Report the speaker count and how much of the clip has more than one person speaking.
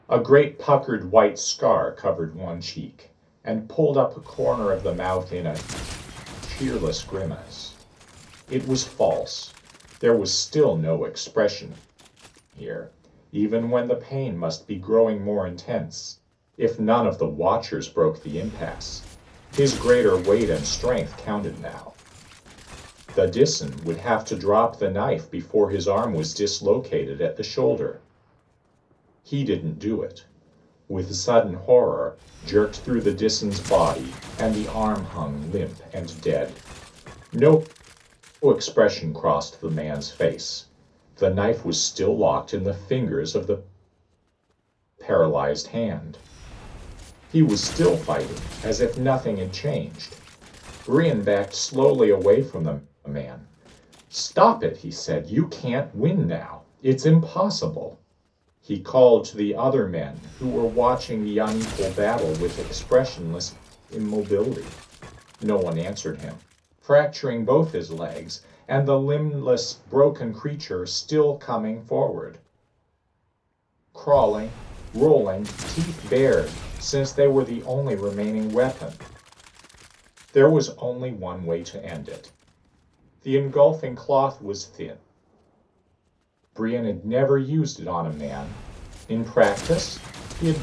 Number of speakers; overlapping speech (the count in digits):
1, no overlap